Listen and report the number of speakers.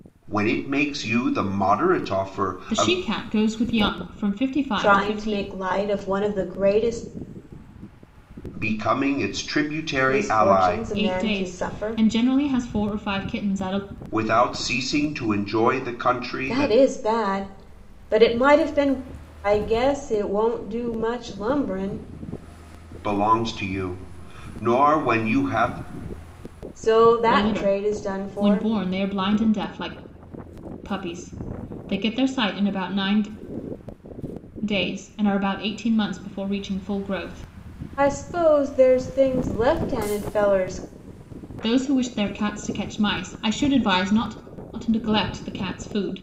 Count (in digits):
3